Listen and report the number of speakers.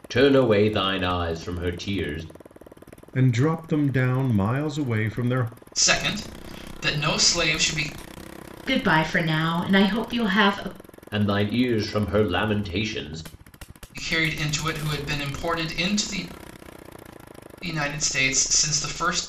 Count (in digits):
4